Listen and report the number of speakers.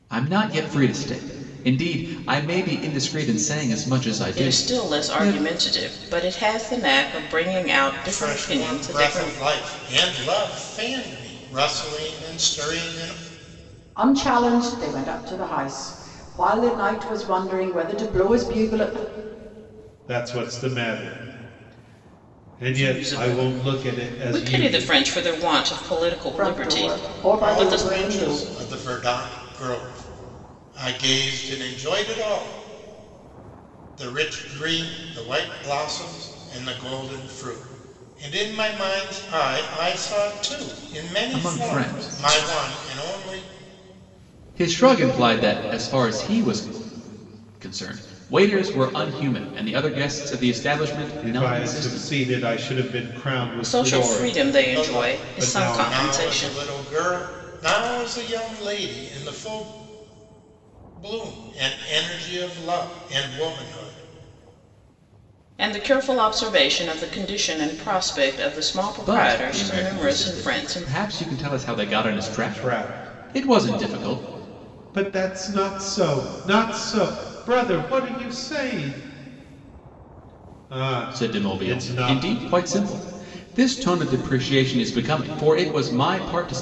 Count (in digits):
5